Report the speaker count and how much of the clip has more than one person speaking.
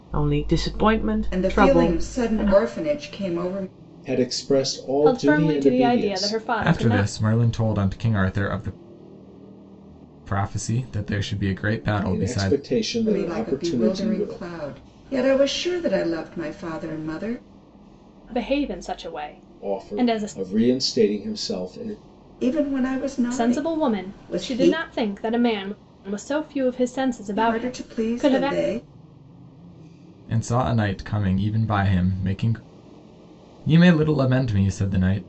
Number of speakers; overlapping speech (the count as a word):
five, about 24%